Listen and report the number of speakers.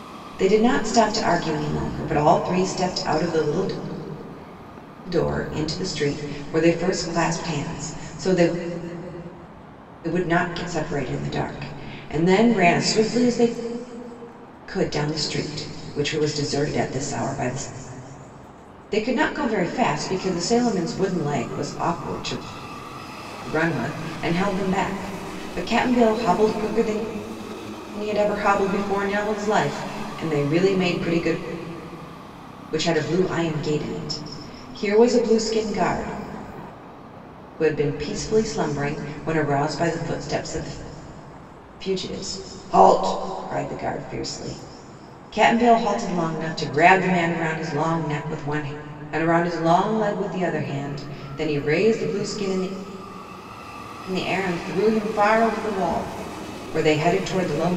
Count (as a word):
one